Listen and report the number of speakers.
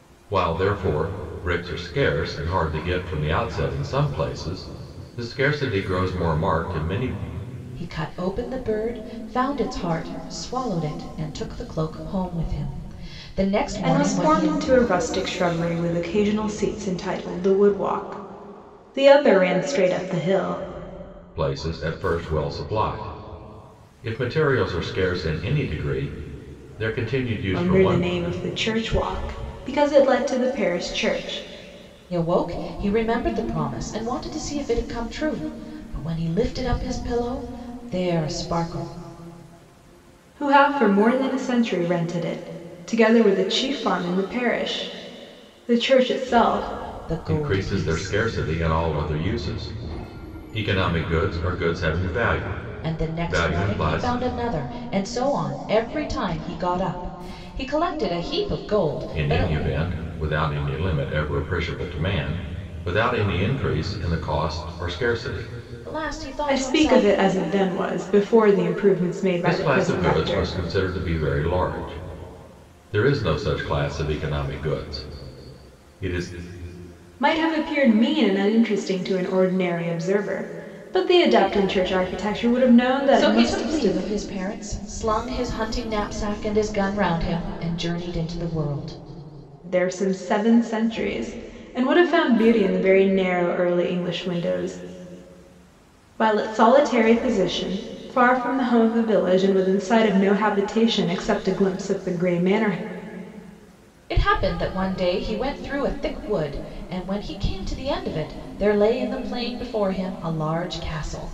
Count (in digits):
3